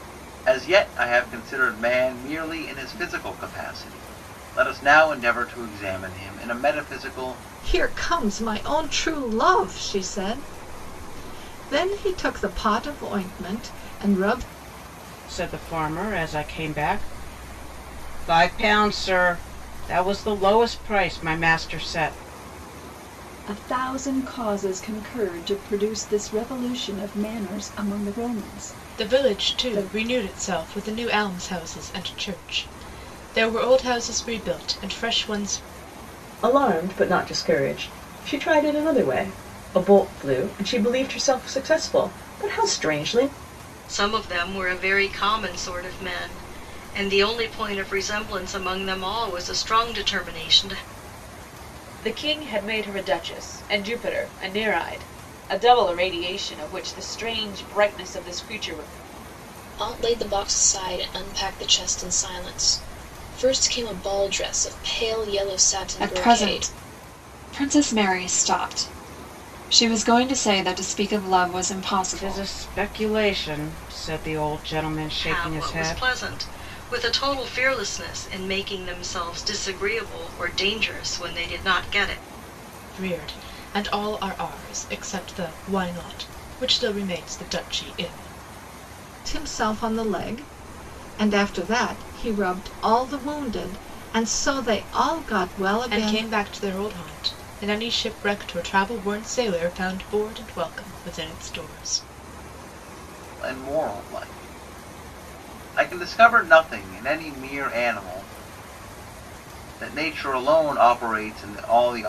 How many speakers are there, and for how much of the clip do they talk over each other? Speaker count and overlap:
10, about 3%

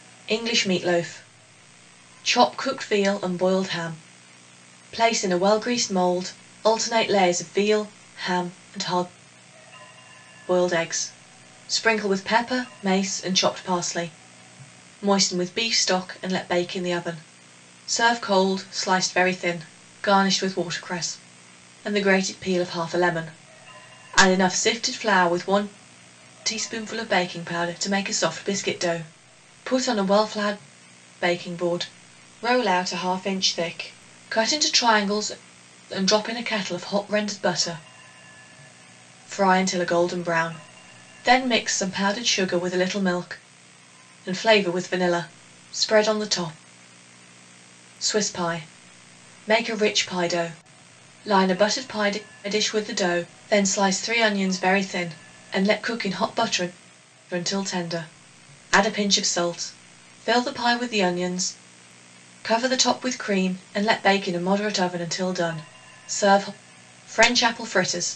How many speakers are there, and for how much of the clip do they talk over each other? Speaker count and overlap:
1, no overlap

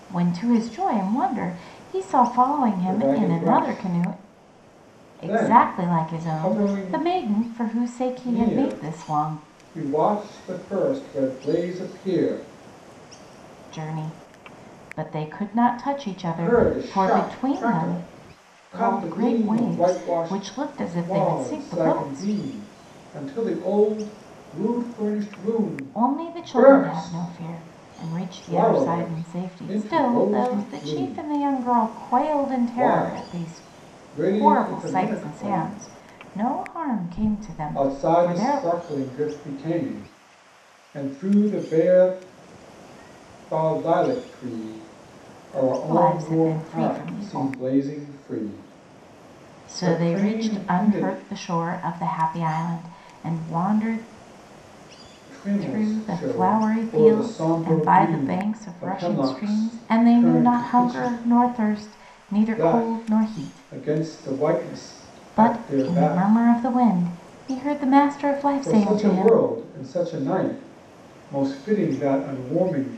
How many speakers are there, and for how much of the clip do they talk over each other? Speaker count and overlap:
2, about 39%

